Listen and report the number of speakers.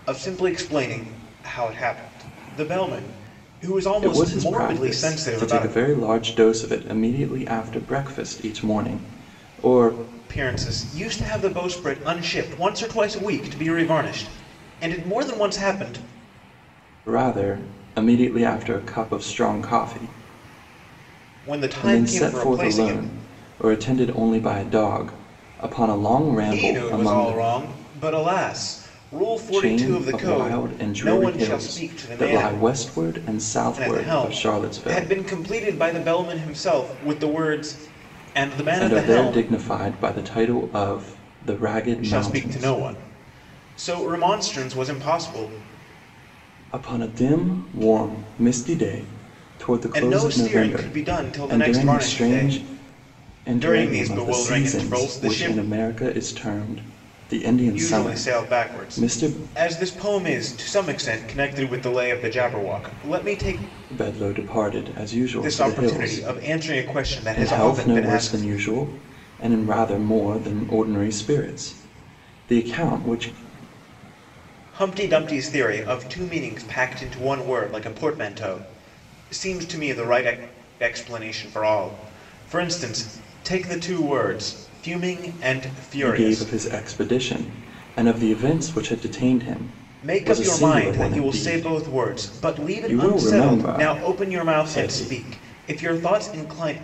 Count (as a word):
two